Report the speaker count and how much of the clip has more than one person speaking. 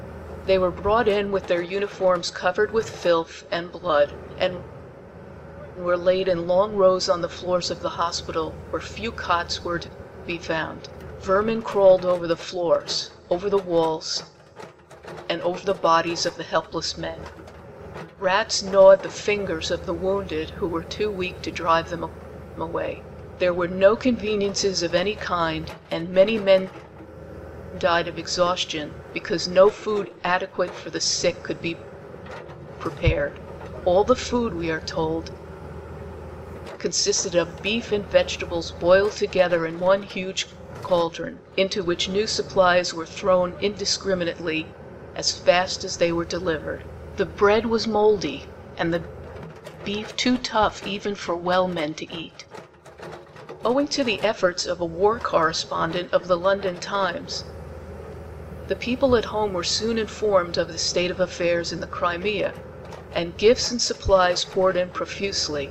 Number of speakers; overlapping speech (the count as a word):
one, no overlap